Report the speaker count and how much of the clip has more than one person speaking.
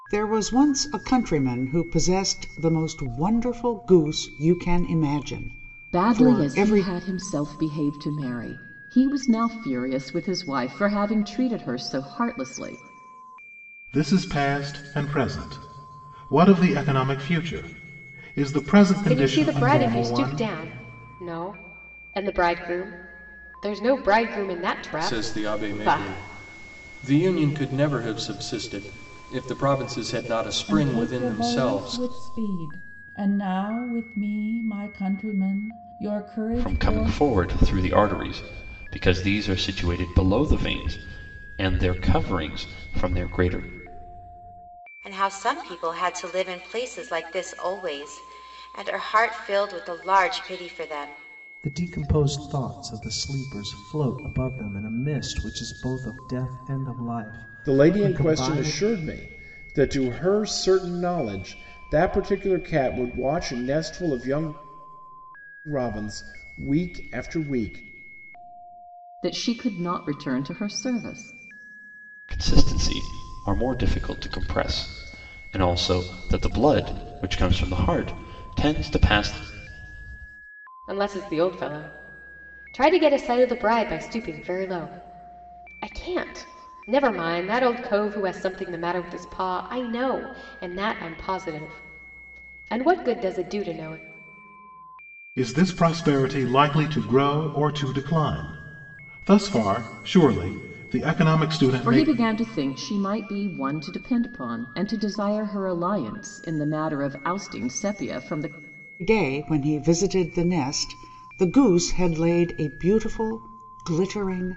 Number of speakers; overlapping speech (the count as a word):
ten, about 6%